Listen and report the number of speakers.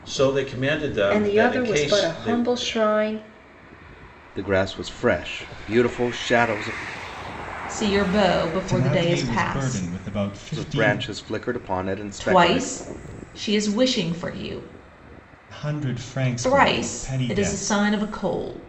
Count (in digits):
5